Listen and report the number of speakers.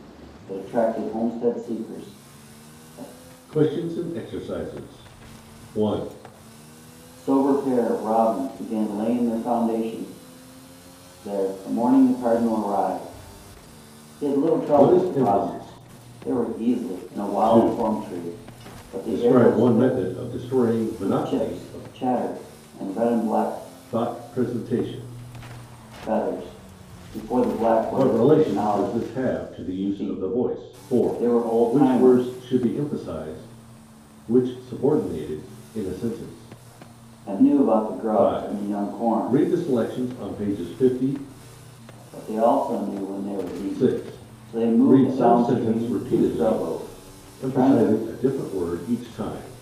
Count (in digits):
2